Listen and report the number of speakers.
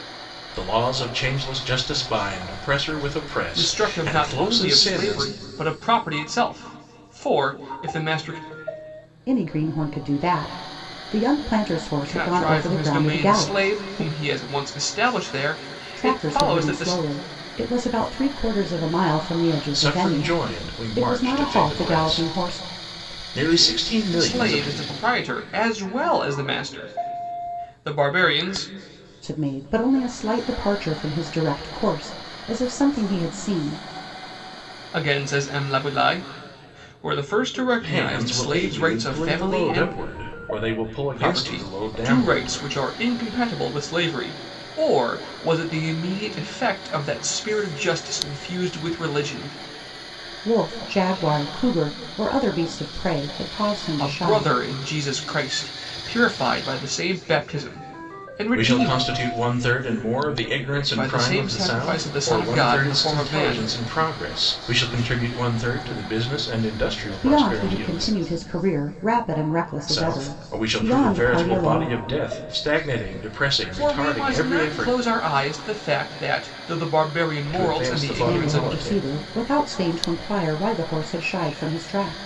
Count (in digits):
3